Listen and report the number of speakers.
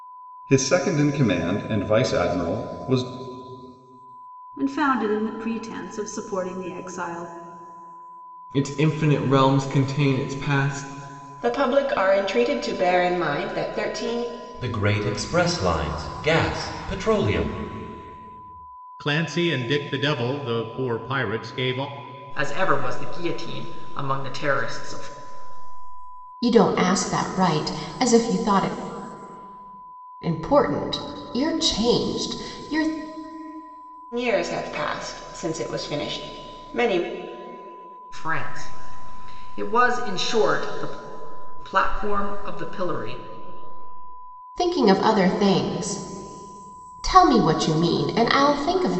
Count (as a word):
eight